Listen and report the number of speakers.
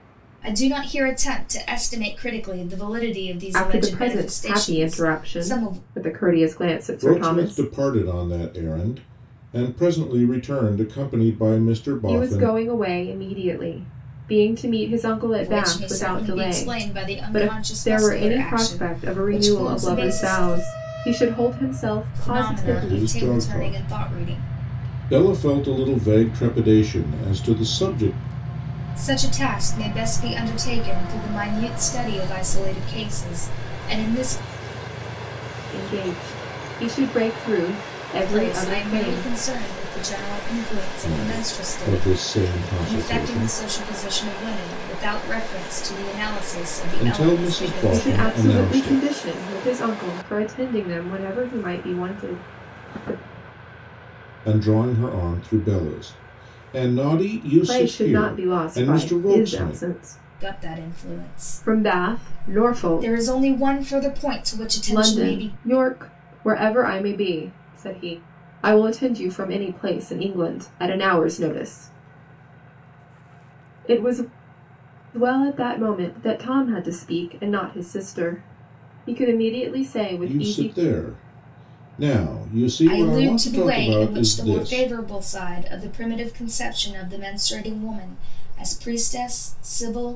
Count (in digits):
3